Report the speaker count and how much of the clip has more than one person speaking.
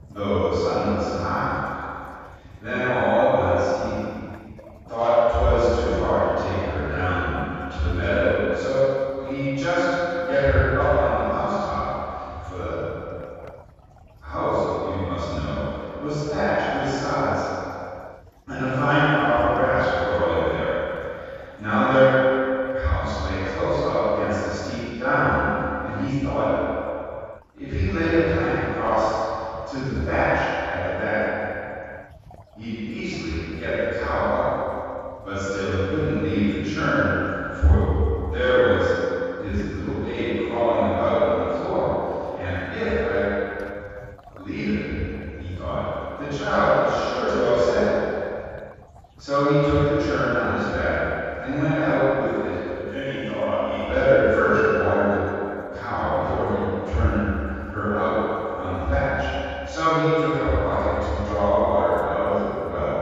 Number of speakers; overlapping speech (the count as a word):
one, no overlap